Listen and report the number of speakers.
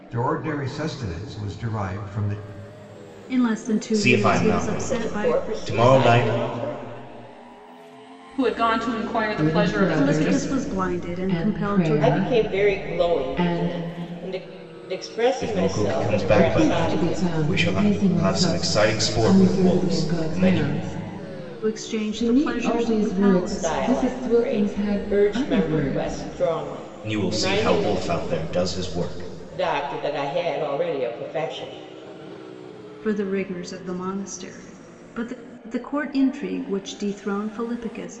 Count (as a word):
six